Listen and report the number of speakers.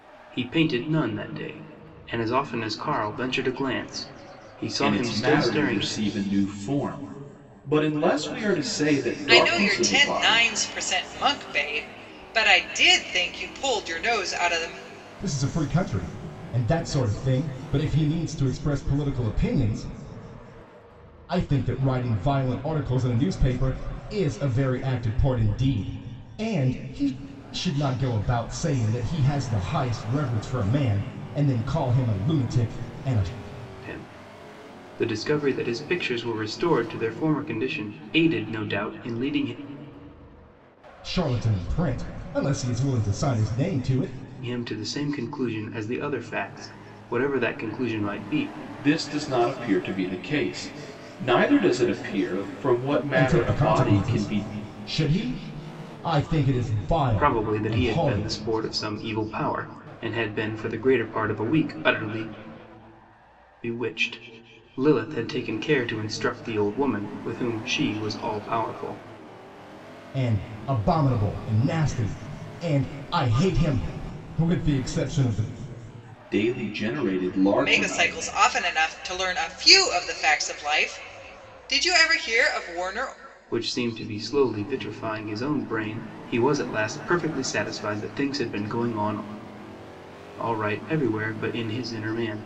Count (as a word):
four